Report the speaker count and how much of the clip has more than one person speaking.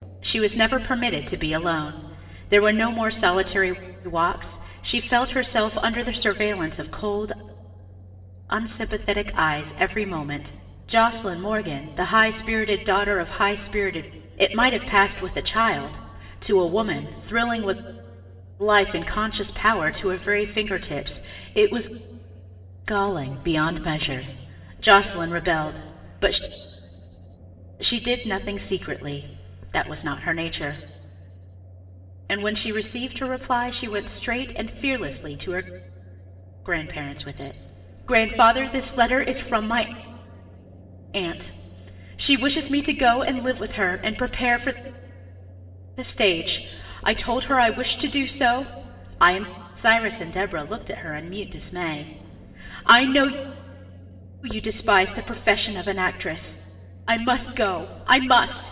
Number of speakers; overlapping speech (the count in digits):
1, no overlap